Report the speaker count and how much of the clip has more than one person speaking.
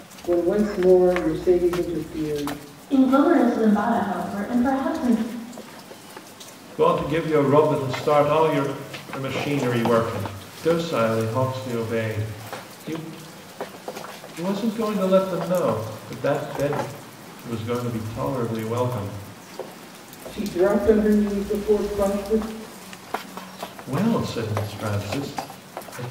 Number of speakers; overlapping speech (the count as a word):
three, no overlap